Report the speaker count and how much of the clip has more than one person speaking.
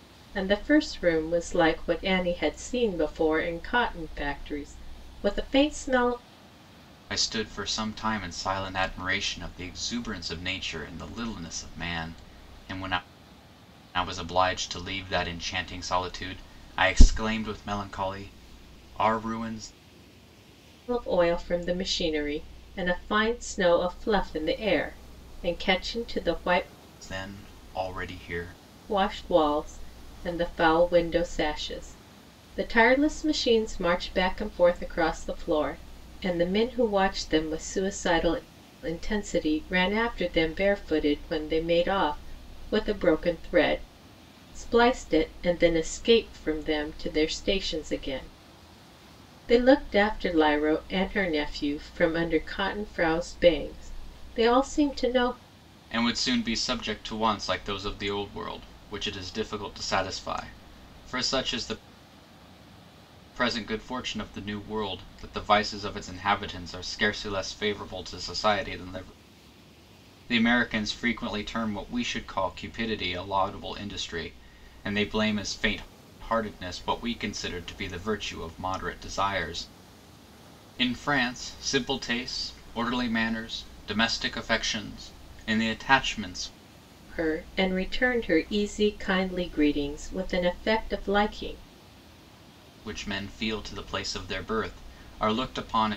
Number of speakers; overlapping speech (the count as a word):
two, no overlap